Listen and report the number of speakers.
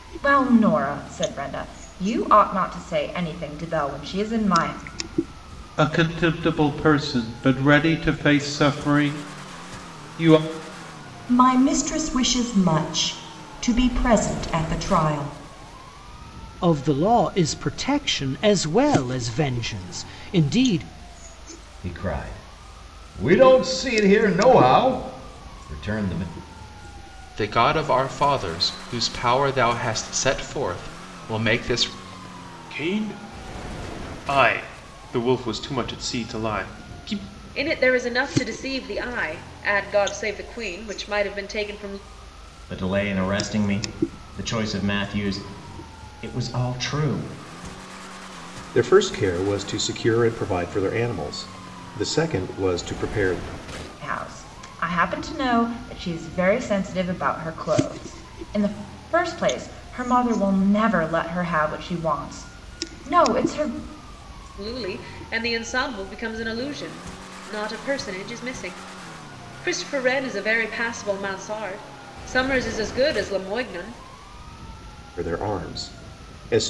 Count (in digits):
10